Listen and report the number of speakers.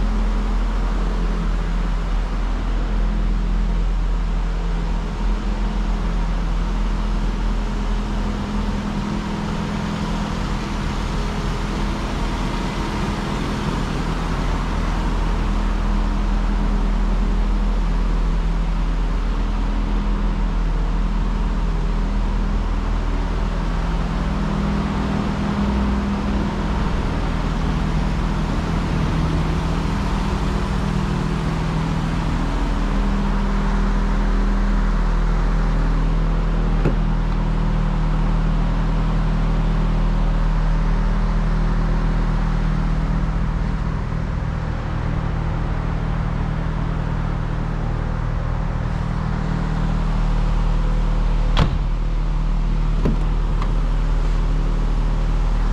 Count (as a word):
zero